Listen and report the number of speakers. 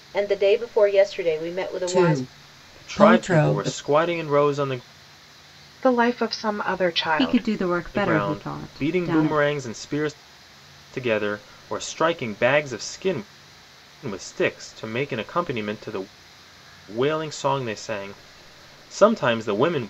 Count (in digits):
5